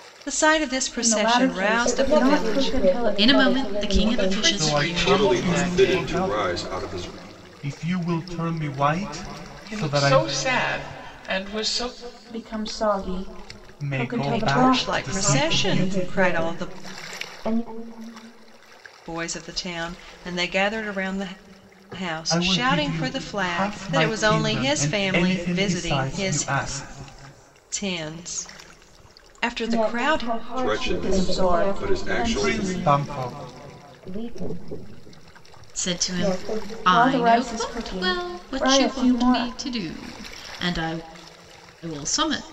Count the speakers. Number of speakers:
7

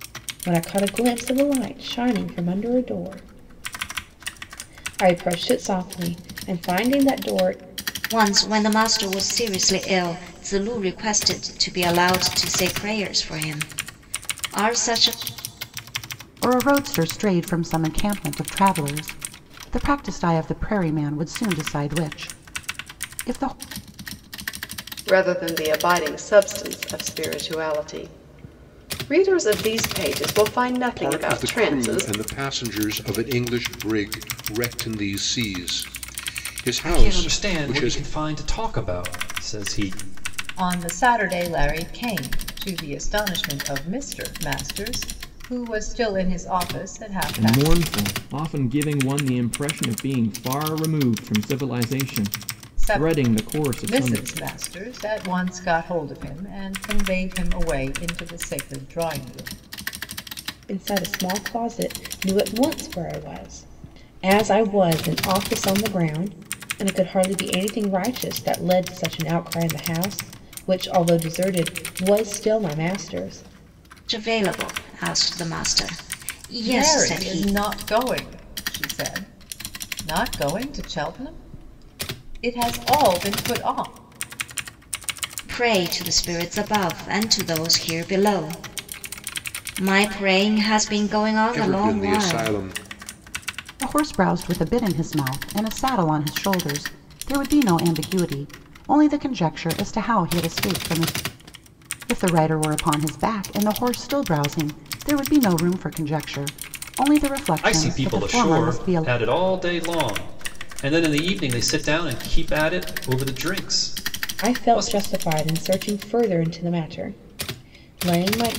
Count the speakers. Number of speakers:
8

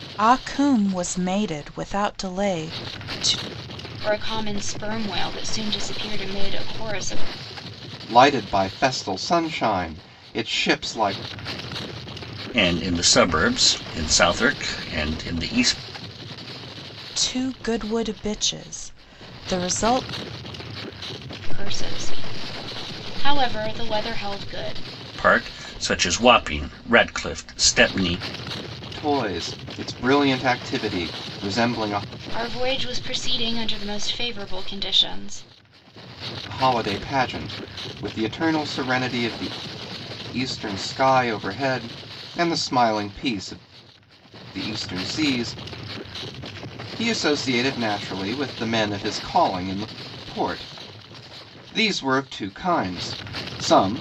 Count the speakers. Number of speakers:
4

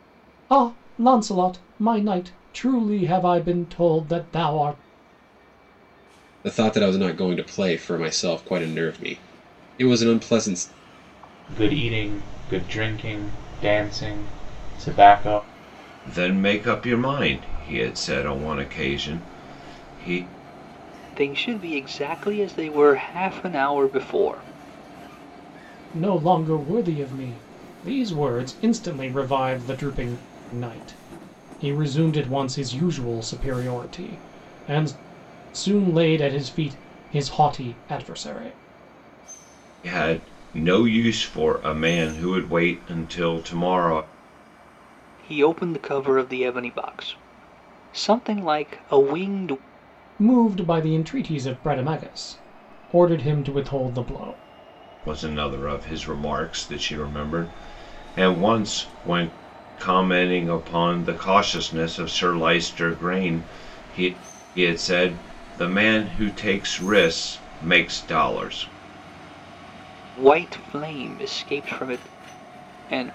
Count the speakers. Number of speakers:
5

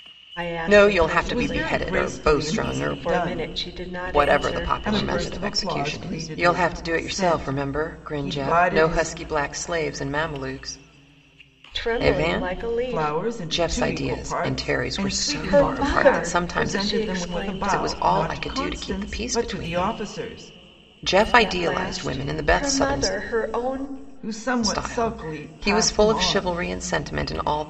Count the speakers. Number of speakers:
3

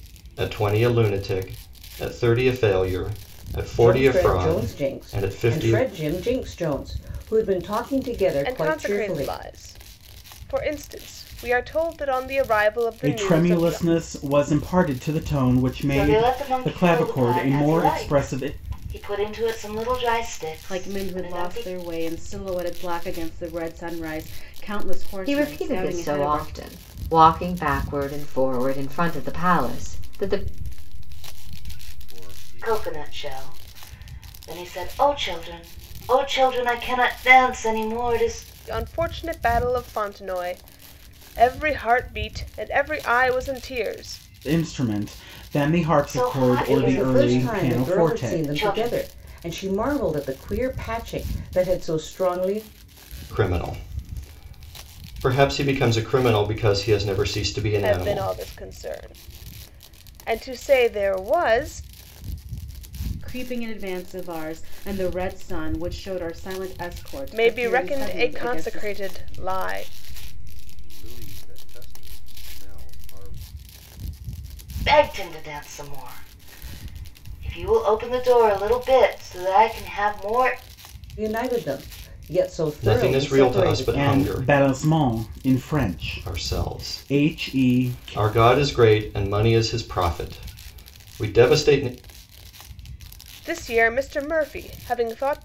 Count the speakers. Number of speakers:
8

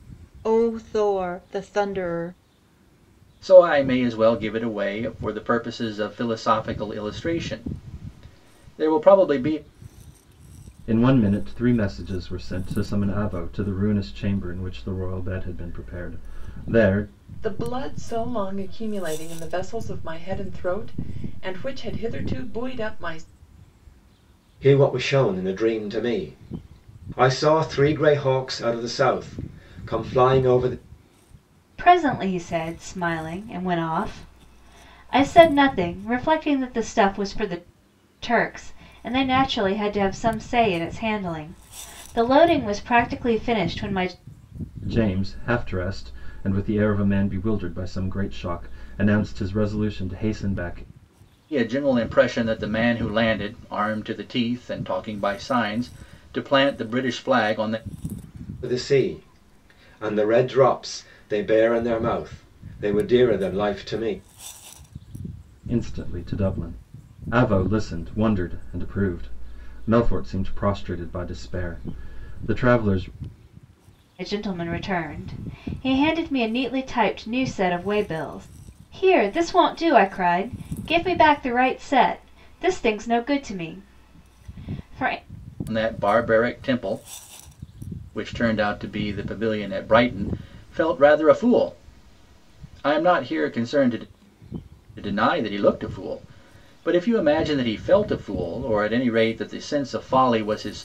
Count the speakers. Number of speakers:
6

